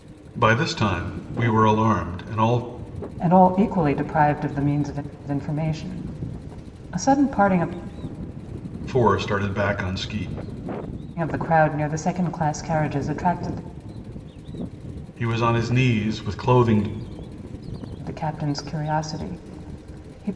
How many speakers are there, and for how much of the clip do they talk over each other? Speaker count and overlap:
2, no overlap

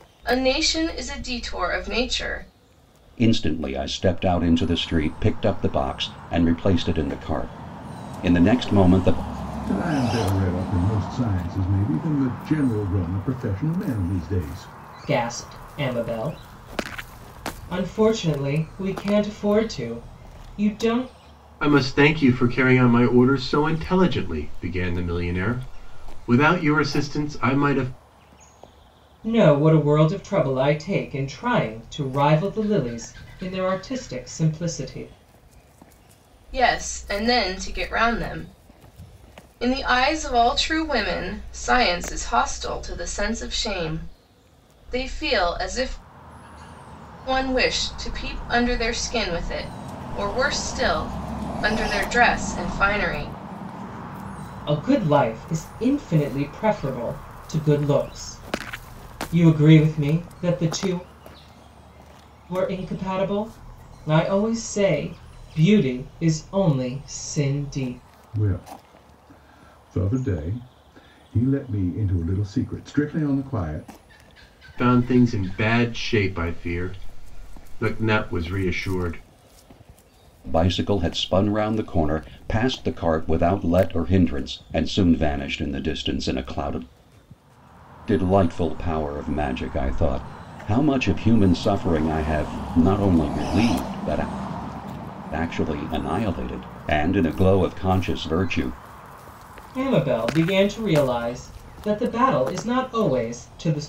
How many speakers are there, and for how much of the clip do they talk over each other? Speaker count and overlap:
5, no overlap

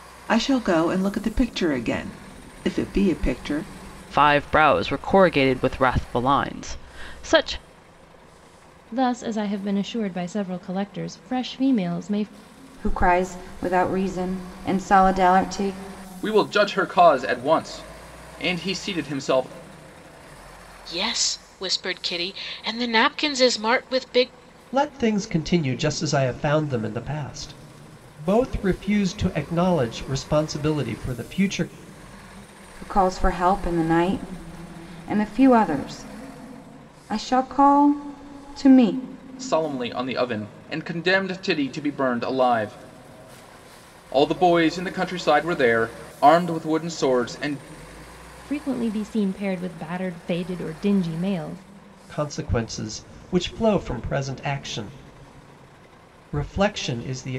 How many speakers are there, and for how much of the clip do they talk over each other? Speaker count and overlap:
7, no overlap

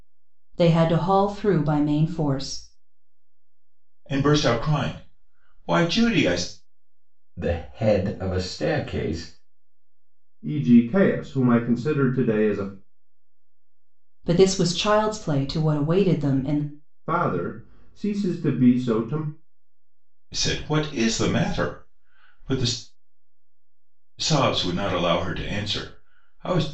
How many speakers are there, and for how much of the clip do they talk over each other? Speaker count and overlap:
4, no overlap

